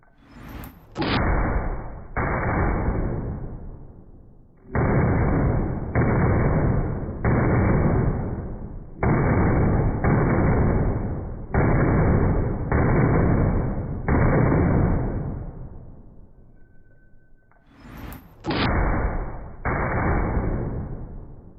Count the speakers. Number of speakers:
0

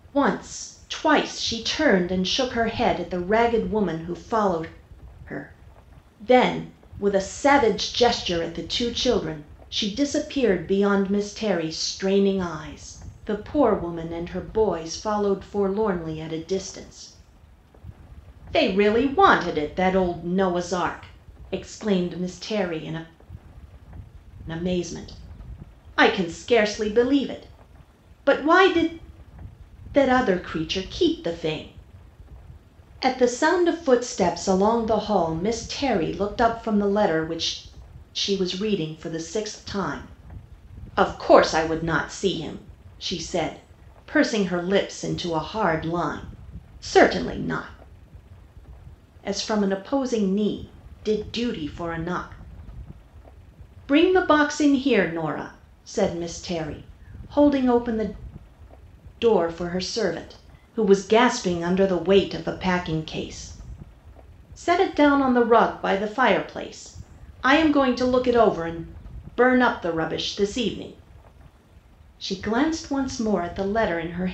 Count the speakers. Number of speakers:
1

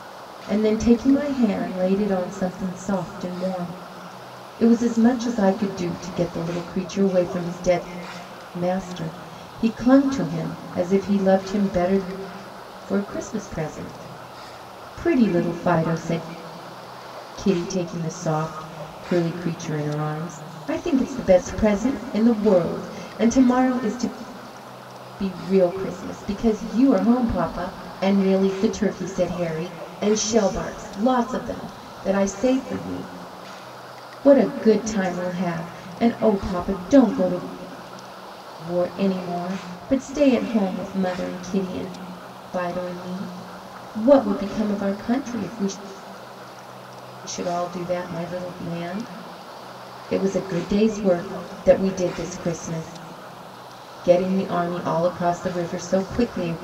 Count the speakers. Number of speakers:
1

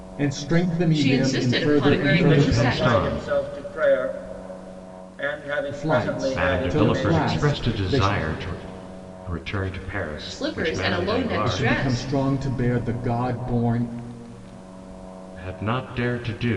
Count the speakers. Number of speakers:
4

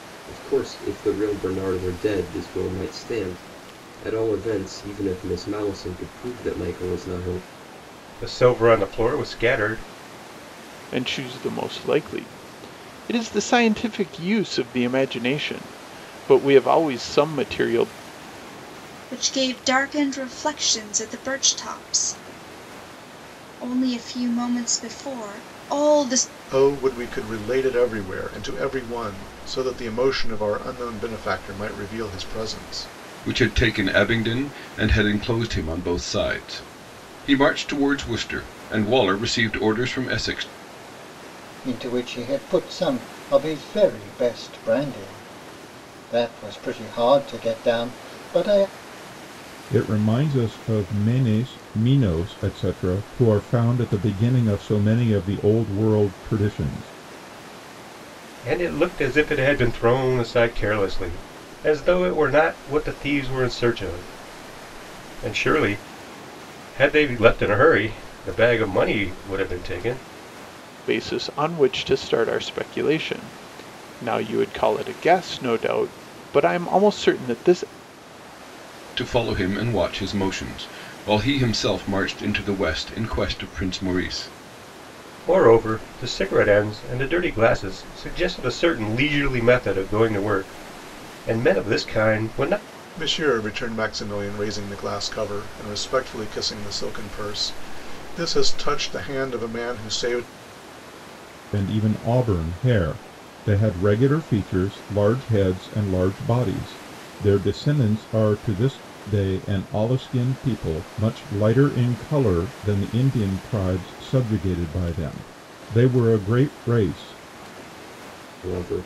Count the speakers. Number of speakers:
8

